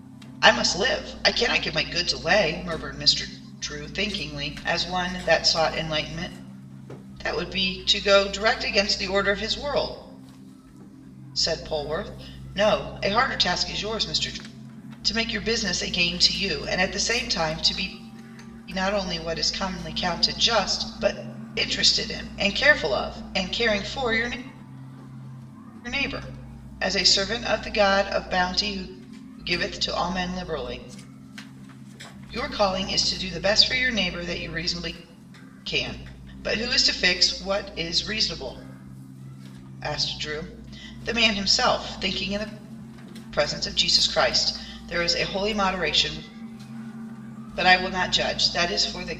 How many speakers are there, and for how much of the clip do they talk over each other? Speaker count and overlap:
1, no overlap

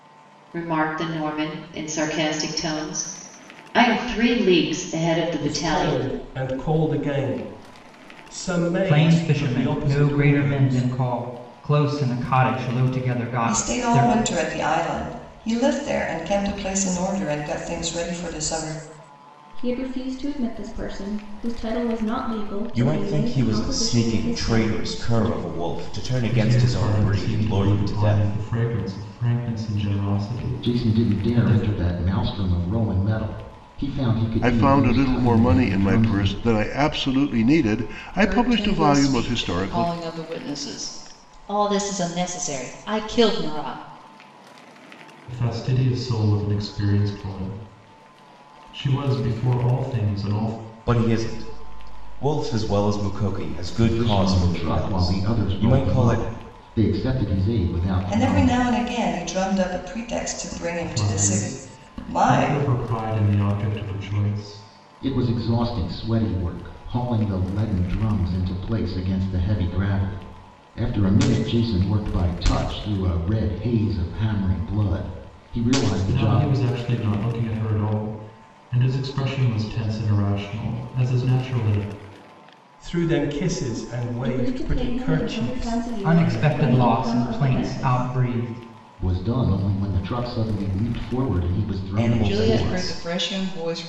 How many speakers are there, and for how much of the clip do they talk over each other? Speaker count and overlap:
10, about 25%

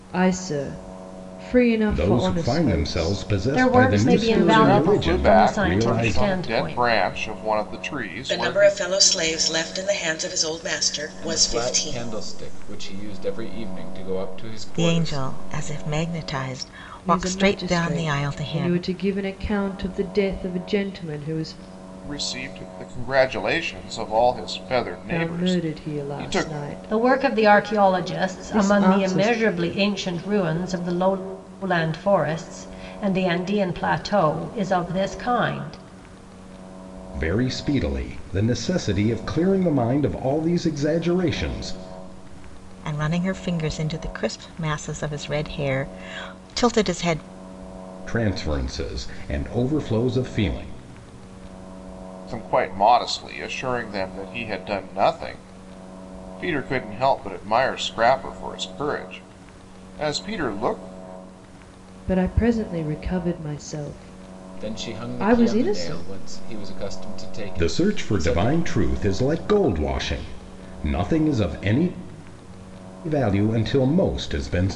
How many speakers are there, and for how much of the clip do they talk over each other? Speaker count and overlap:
7, about 21%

